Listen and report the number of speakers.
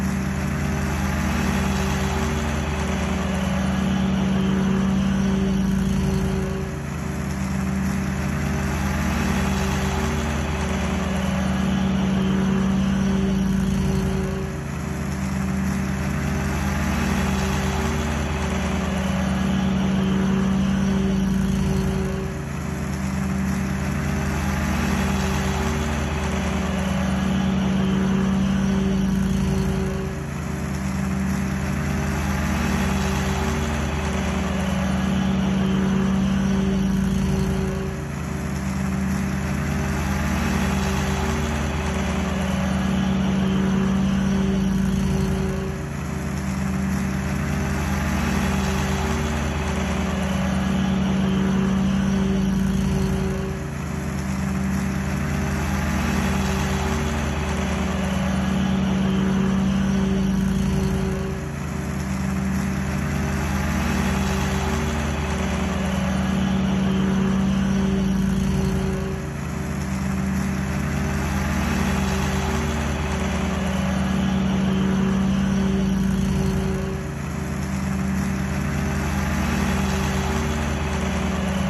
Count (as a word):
zero